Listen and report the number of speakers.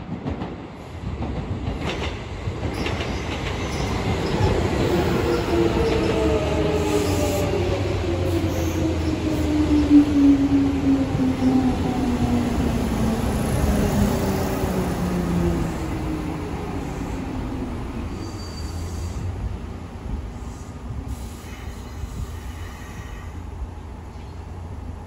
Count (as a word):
zero